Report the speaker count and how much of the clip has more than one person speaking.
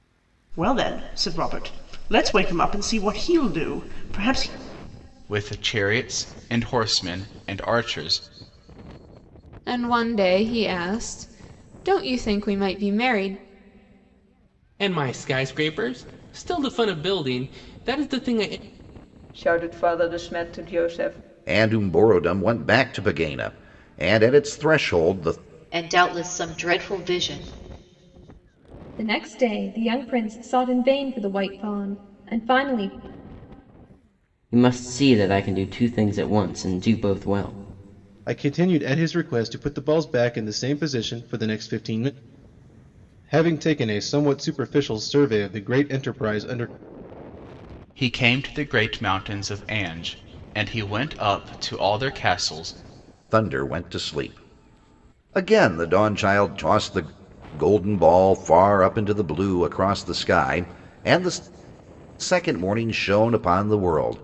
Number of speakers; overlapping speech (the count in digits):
10, no overlap